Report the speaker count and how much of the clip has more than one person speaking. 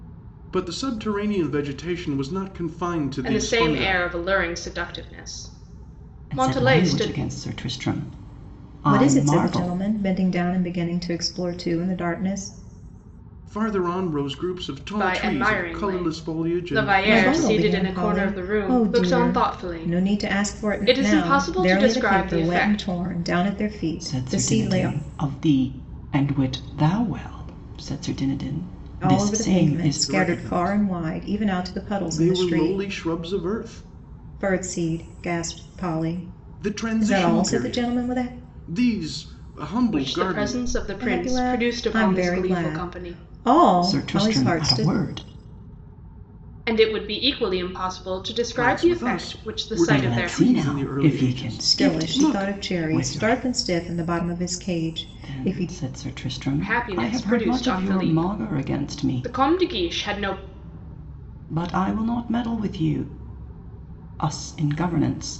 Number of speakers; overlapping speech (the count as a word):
four, about 45%